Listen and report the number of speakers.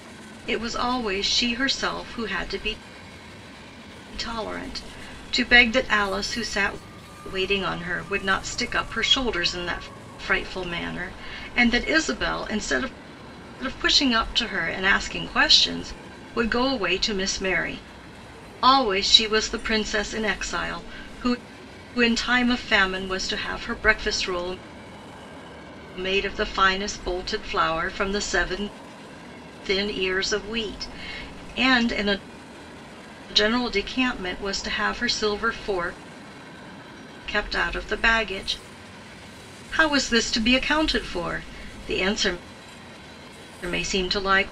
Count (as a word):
one